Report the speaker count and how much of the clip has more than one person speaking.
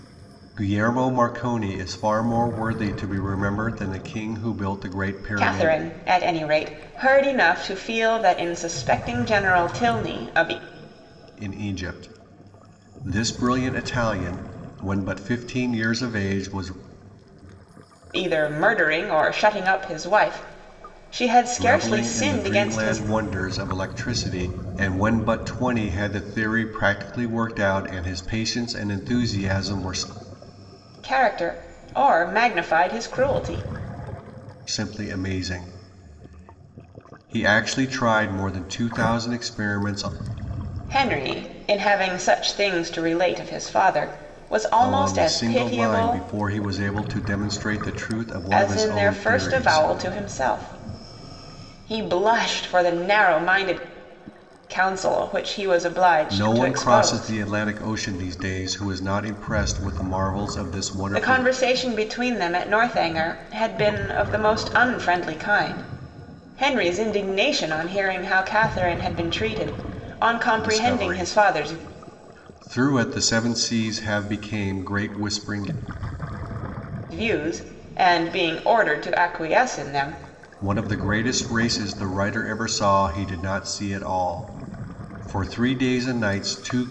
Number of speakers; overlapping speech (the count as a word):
two, about 9%